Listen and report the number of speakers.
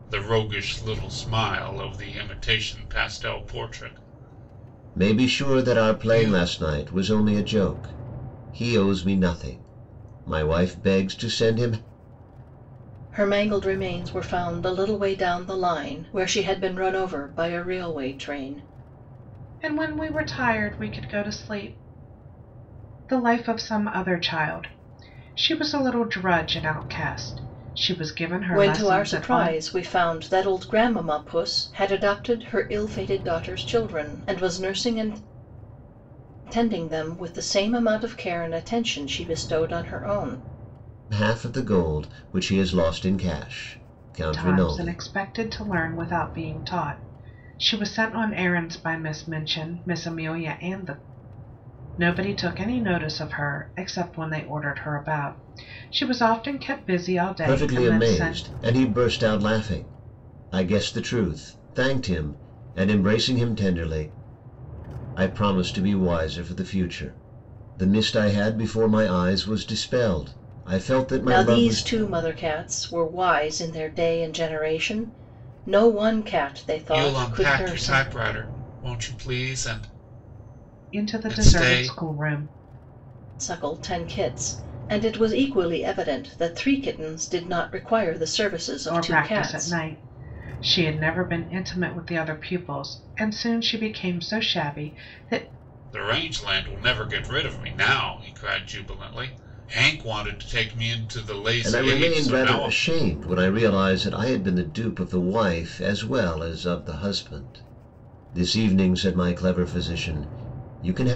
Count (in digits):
4